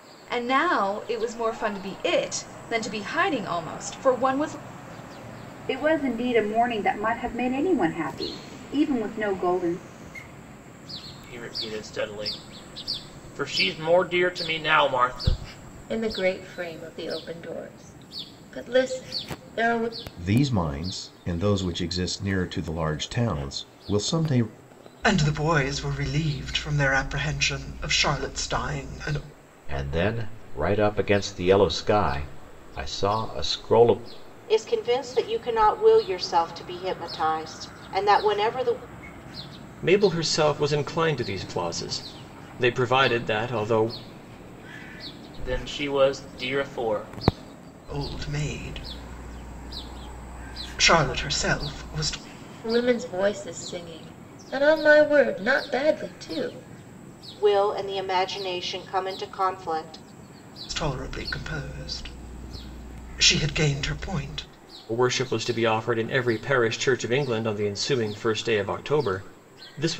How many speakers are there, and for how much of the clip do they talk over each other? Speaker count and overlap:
nine, no overlap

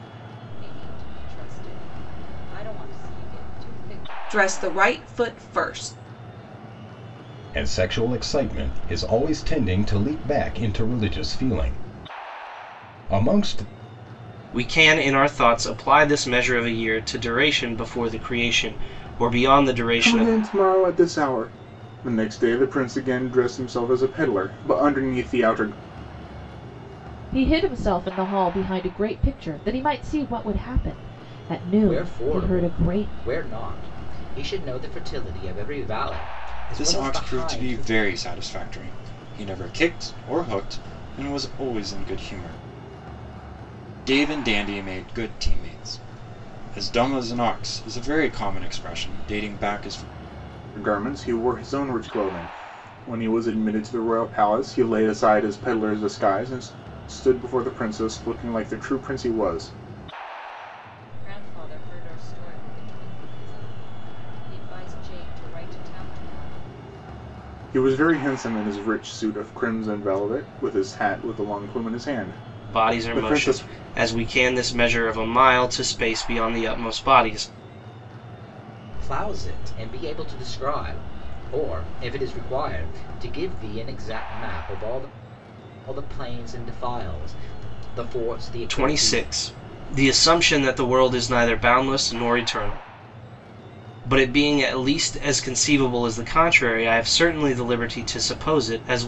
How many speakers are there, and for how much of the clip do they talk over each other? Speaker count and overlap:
eight, about 5%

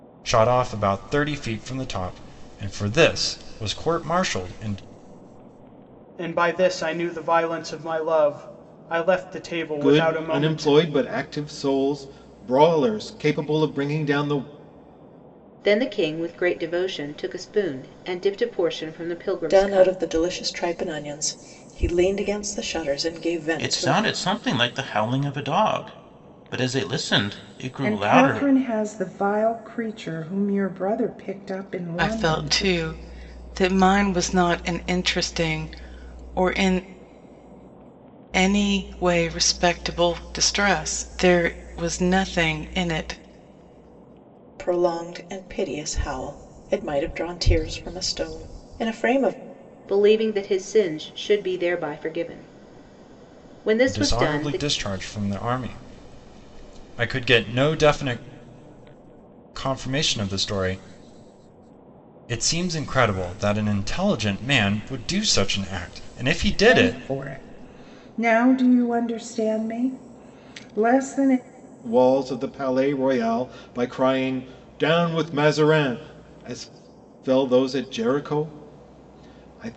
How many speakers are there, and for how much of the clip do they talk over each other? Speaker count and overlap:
eight, about 6%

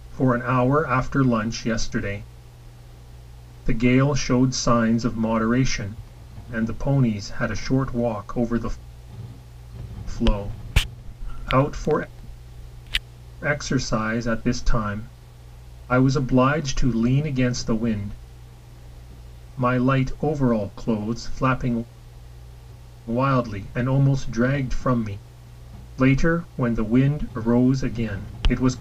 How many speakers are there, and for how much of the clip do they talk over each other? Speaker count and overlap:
one, no overlap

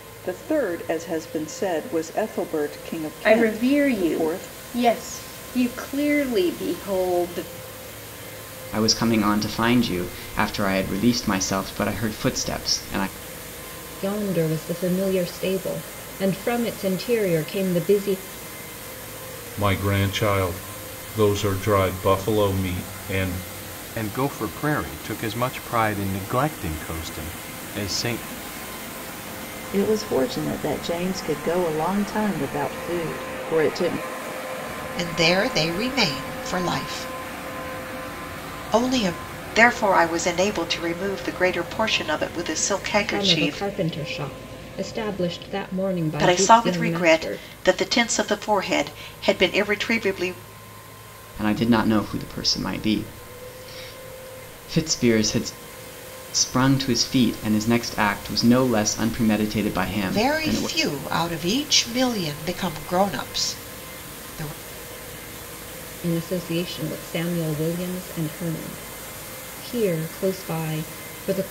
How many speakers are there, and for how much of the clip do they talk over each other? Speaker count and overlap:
nine, about 5%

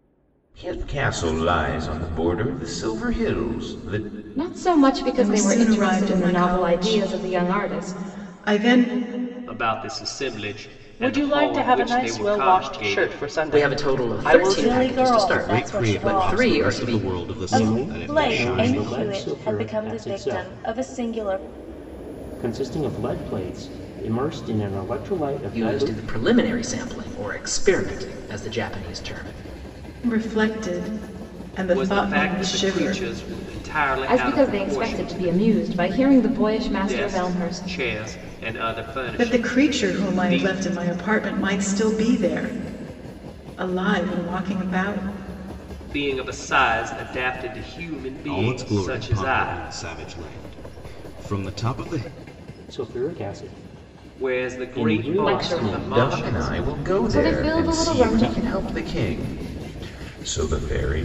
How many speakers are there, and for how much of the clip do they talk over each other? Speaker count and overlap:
nine, about 39%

